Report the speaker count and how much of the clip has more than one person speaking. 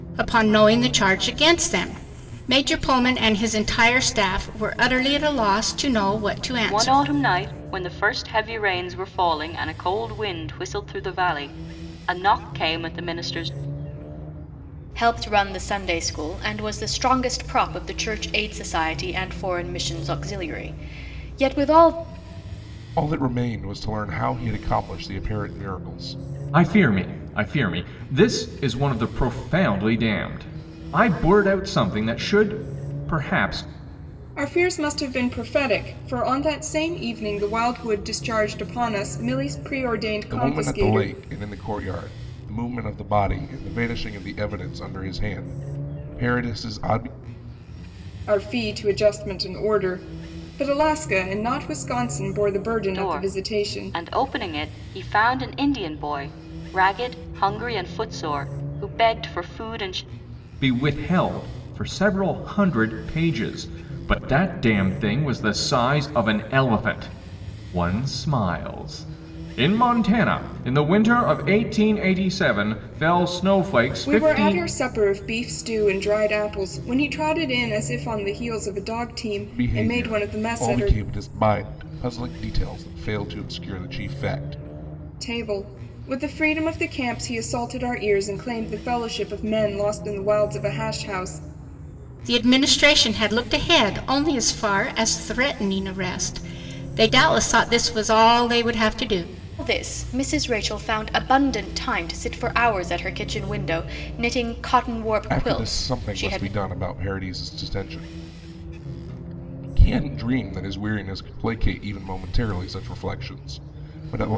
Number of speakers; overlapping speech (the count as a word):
six, about 5%